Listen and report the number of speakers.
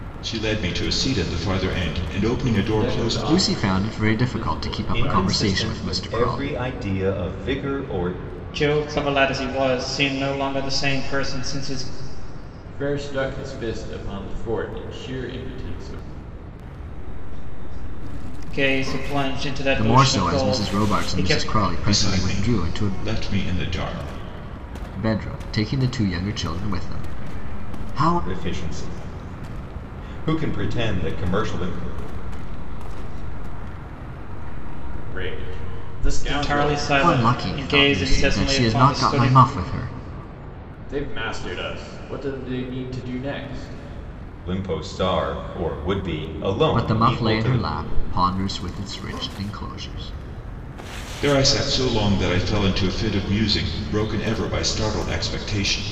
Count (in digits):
6